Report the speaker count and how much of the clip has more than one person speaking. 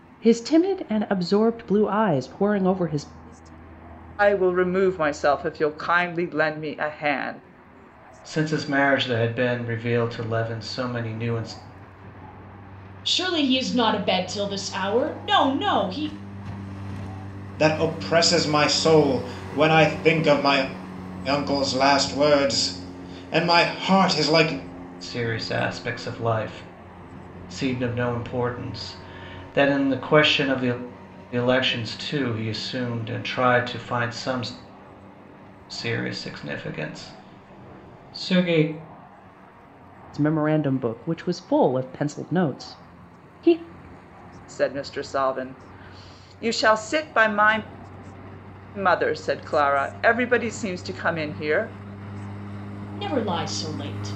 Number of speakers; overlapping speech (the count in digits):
5, no overlap